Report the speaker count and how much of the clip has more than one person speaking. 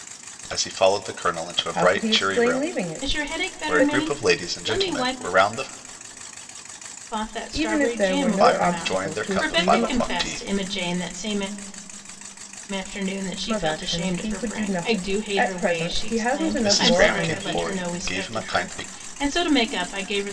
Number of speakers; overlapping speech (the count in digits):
3, about 57%